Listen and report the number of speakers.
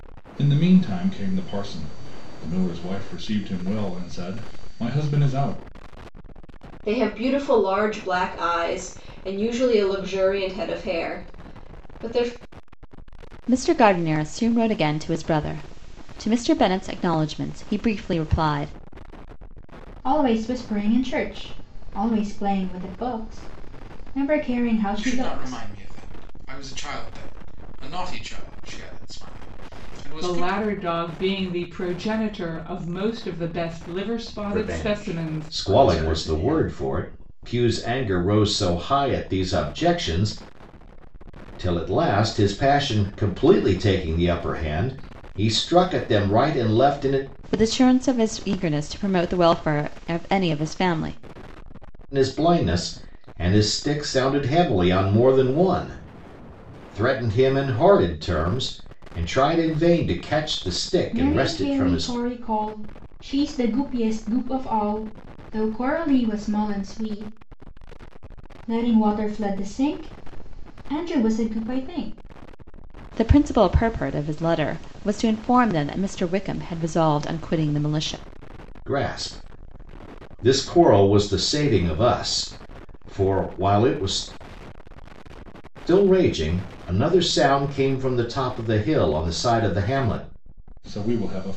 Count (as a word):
eight